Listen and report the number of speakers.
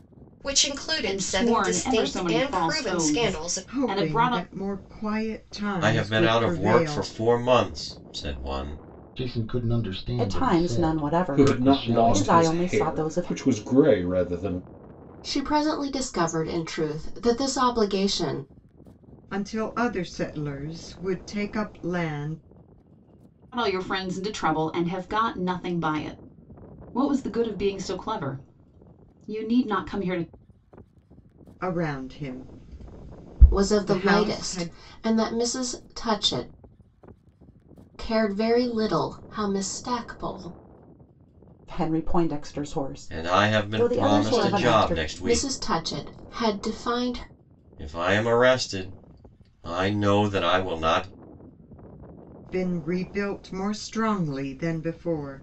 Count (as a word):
eight